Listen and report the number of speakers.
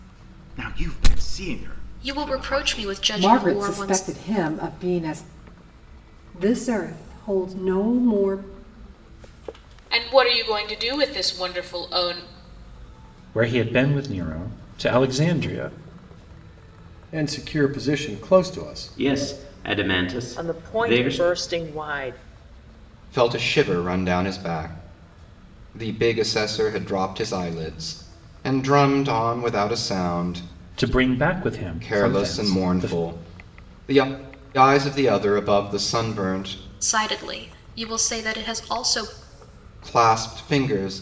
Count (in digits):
10